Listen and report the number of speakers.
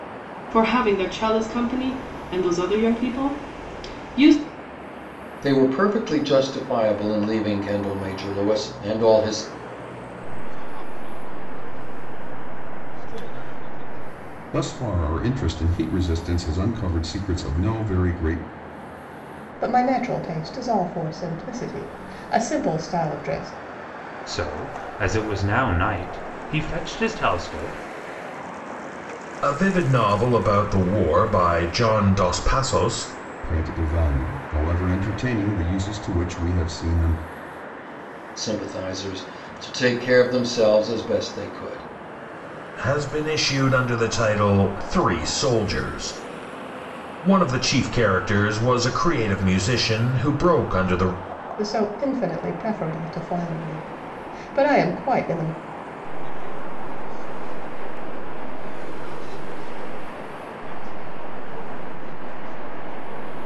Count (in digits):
7